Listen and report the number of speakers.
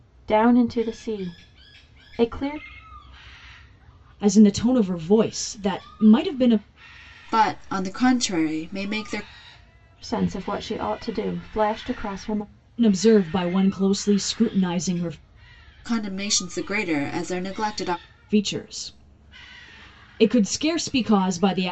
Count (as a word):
three